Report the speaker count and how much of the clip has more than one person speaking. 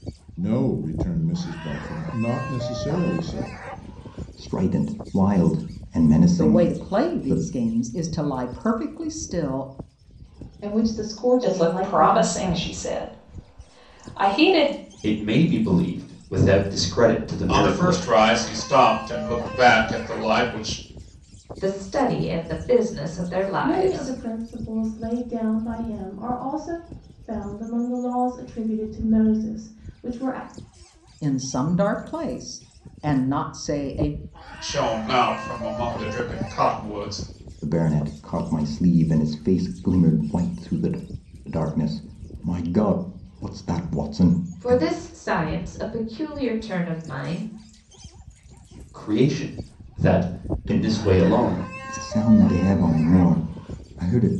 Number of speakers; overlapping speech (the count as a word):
nine, about 9%